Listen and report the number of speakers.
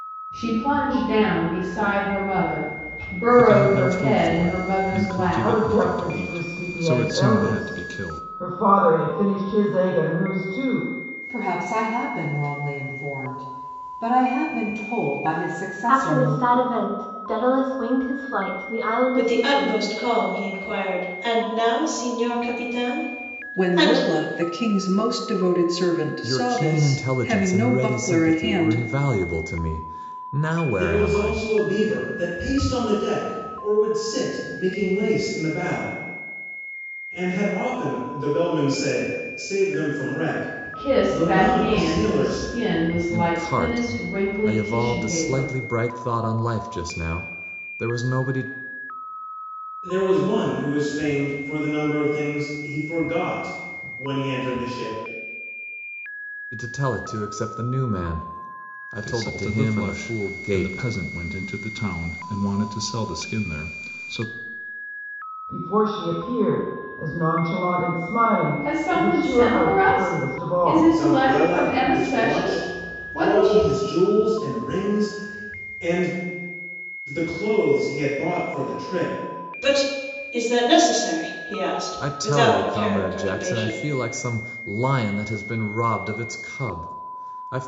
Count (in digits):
9